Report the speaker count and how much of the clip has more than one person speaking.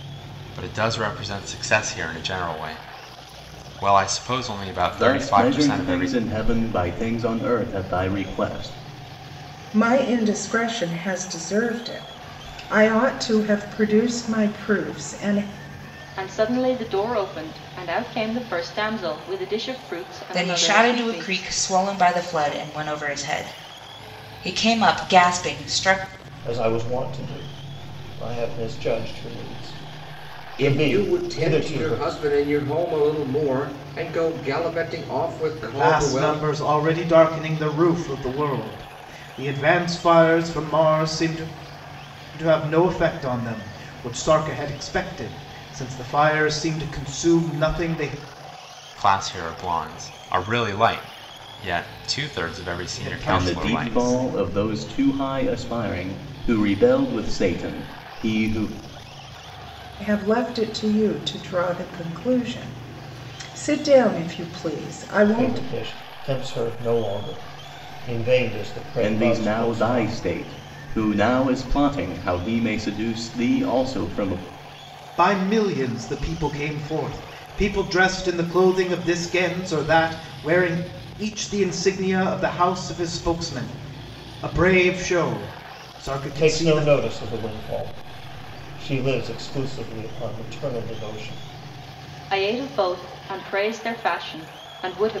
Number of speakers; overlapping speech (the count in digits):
8, about 9%